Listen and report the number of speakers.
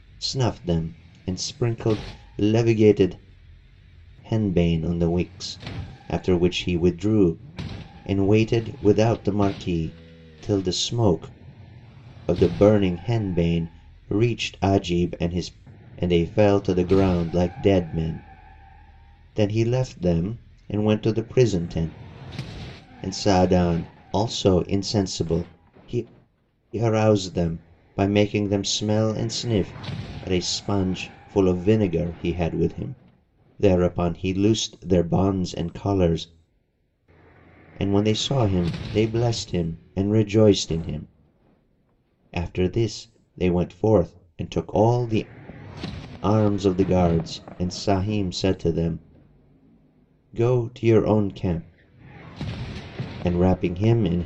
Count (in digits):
1